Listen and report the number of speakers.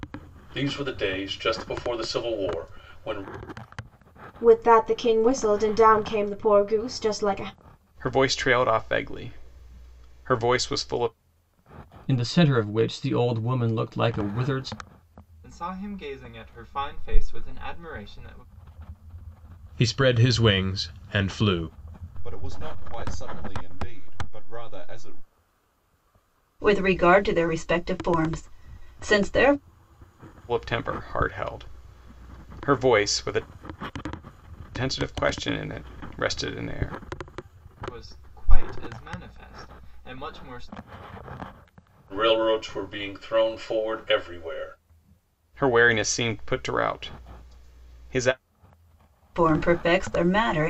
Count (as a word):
eight